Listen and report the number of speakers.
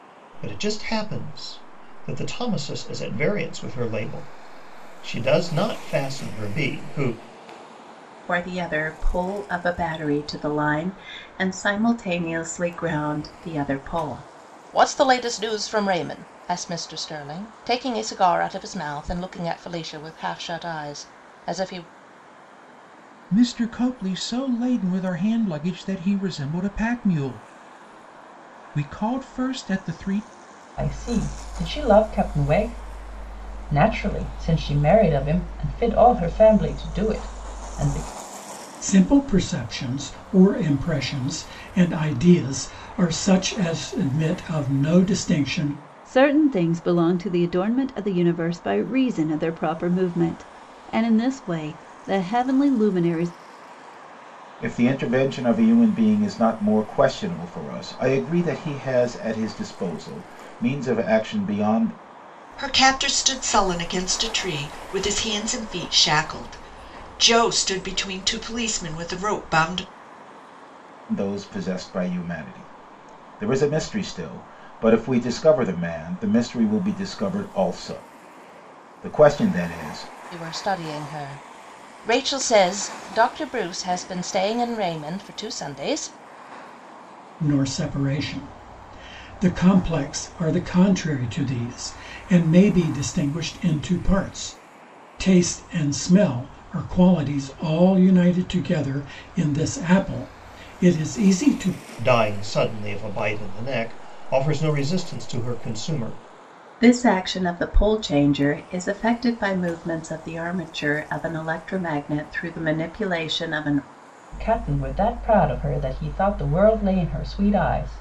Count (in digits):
9